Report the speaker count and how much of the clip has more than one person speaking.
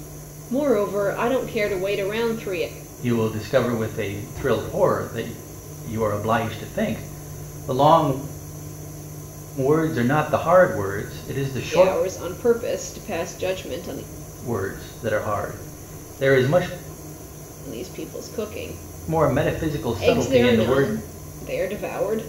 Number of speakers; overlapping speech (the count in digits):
2, about 6%